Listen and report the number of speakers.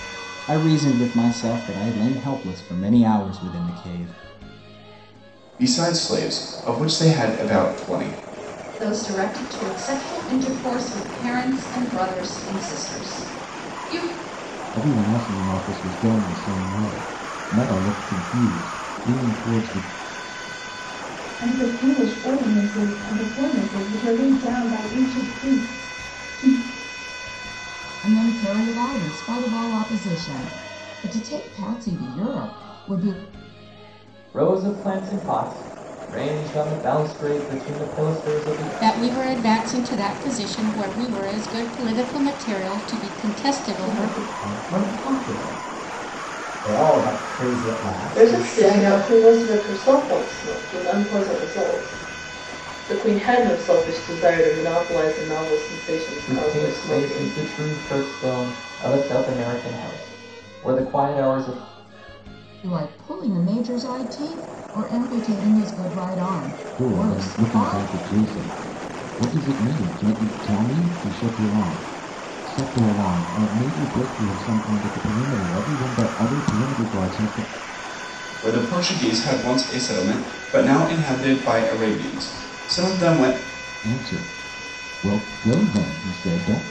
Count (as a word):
ten